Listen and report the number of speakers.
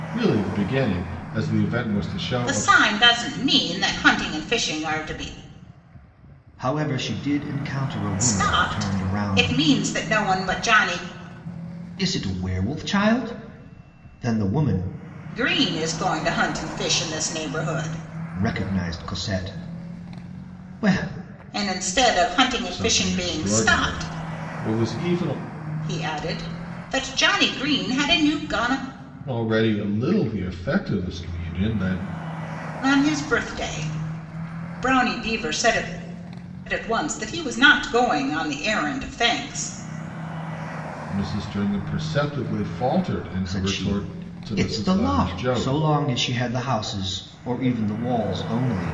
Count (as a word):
three